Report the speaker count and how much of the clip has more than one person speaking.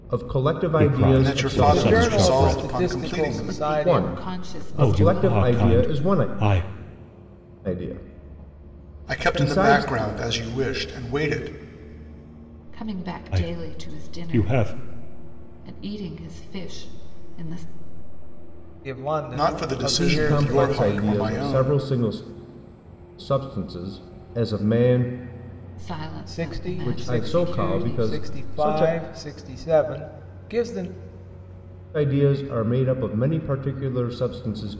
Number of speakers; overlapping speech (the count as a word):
five, about 36%